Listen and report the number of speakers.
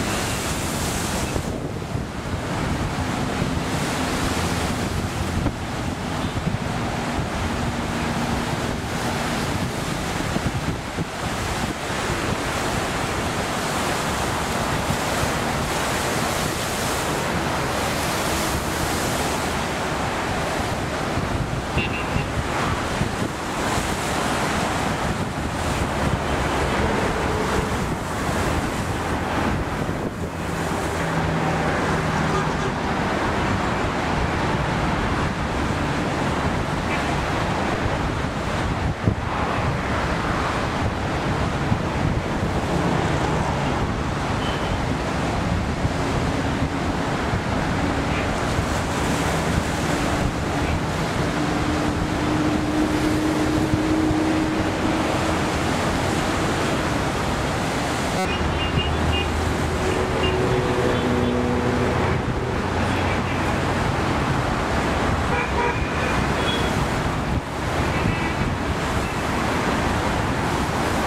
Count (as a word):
zero